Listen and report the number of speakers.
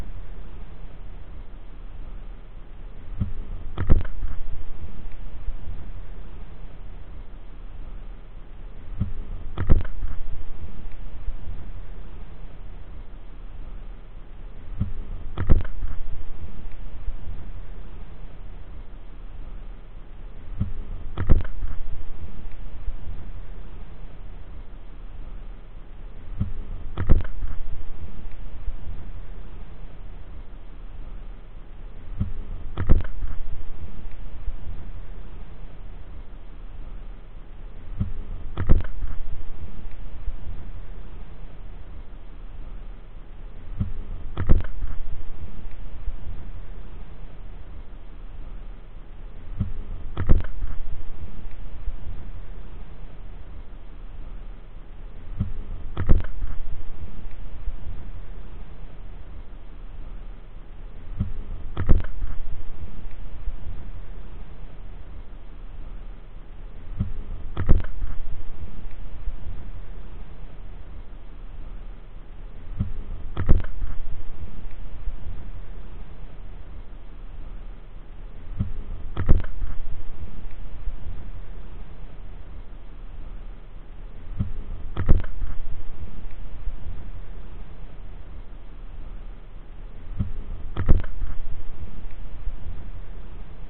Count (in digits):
0